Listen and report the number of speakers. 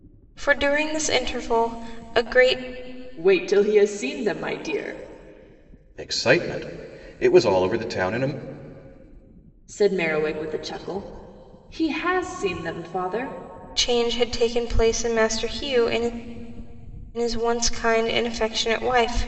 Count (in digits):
3